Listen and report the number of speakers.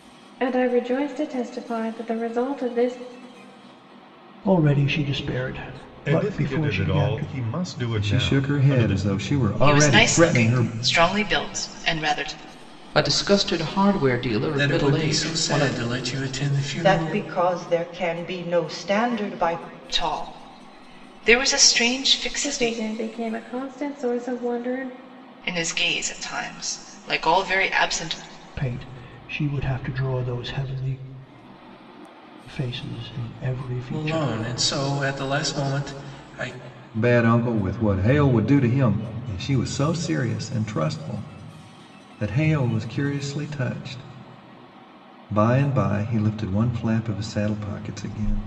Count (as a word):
eight